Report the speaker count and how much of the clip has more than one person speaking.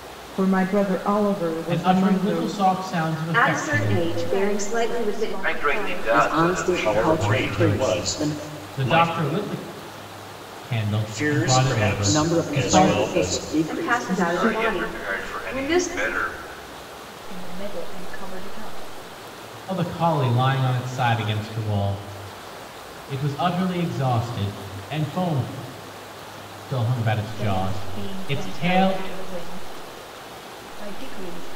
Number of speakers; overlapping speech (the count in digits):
7, about 42%